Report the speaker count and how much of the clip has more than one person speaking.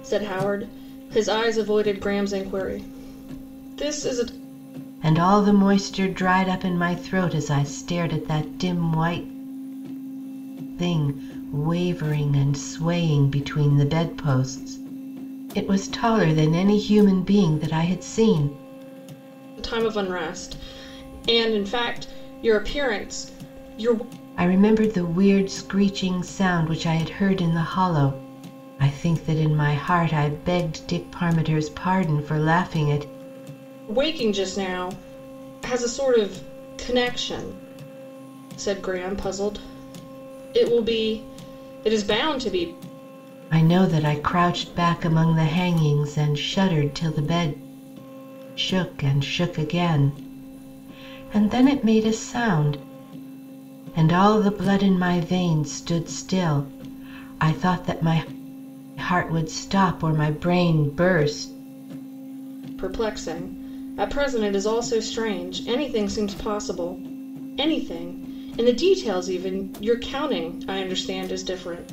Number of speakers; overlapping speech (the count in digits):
2, no overlap